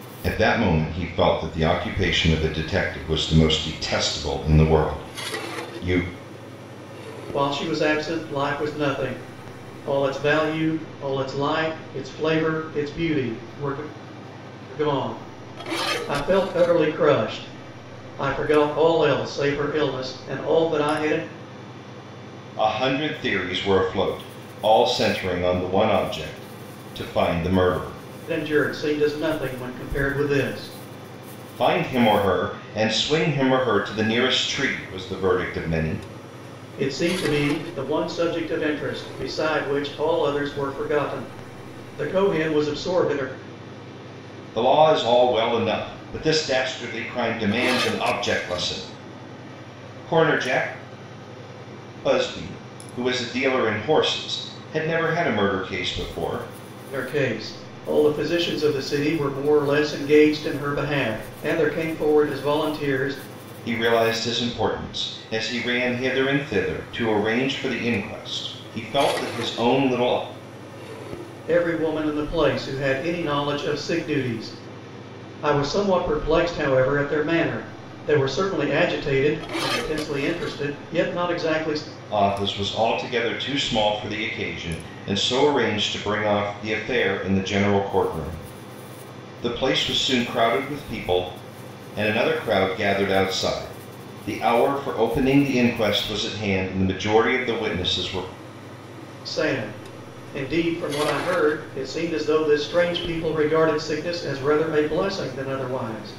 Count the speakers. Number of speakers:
two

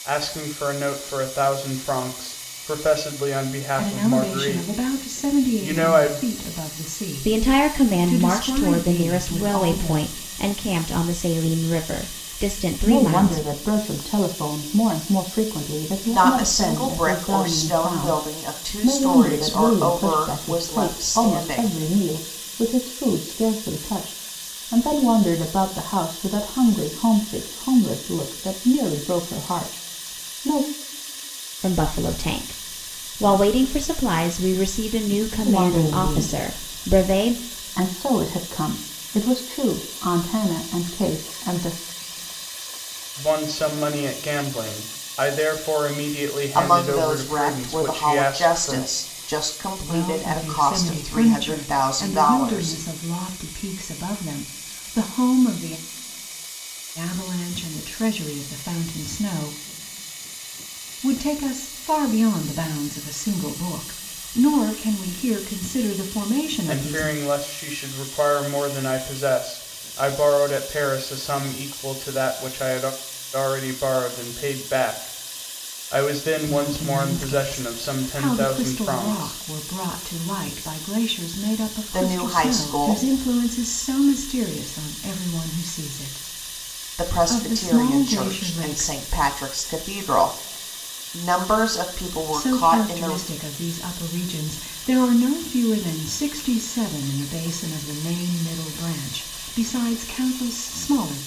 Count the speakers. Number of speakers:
five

